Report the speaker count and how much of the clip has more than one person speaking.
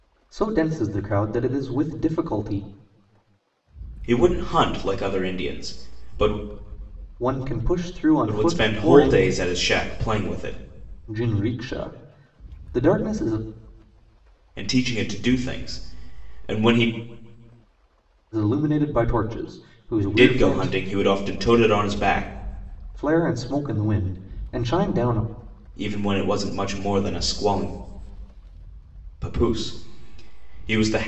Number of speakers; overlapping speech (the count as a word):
two, about 5%